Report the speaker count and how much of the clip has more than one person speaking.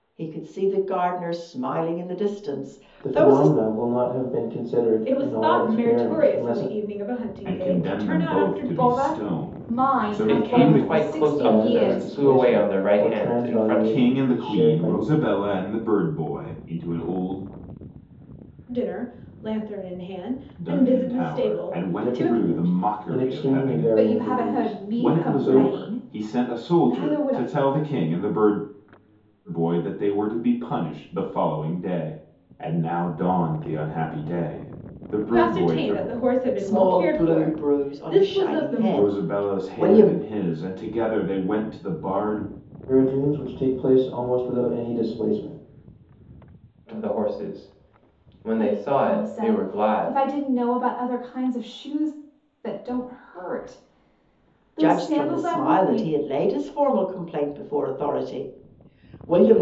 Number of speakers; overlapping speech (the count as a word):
six, about 40%